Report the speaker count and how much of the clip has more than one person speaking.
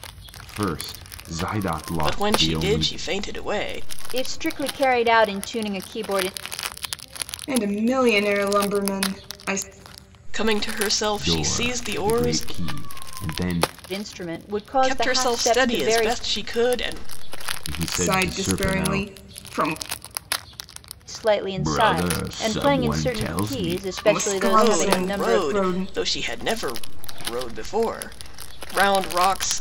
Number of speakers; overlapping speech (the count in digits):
4, about 30%